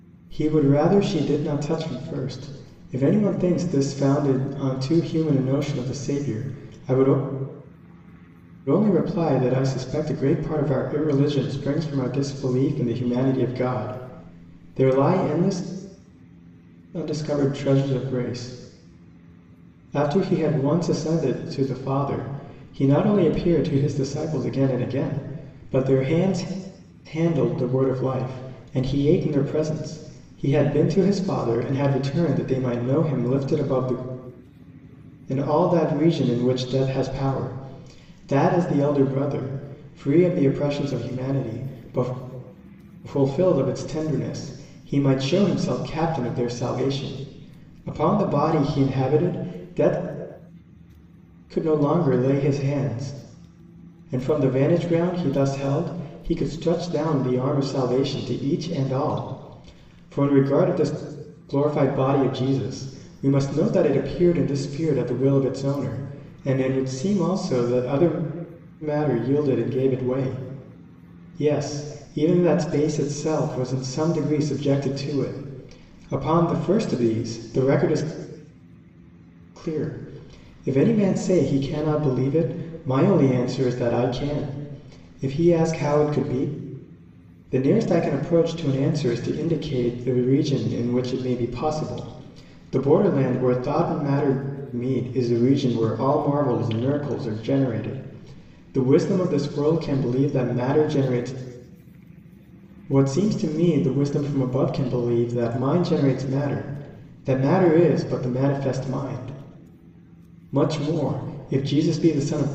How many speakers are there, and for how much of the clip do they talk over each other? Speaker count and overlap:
1, no overlap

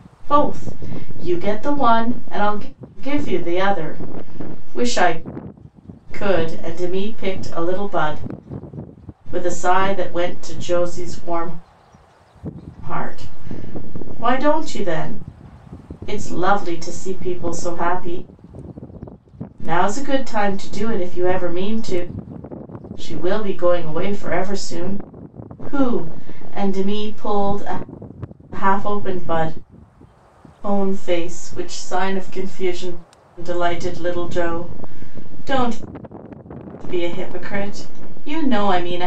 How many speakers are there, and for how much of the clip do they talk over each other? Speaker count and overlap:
1, no overlap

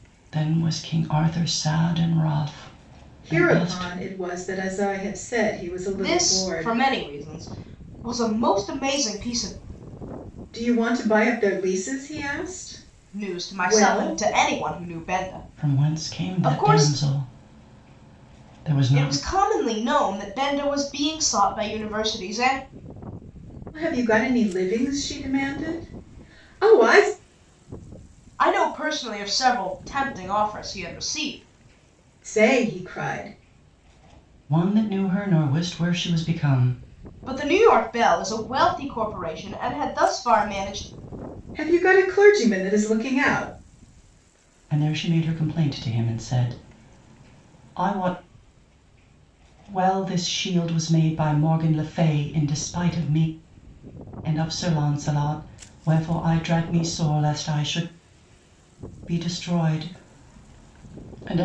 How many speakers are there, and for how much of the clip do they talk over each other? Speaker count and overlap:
3, about 7%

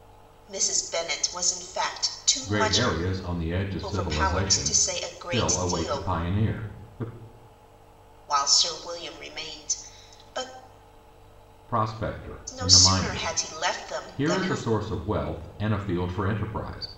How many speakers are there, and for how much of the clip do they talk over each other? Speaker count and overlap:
2, about 22%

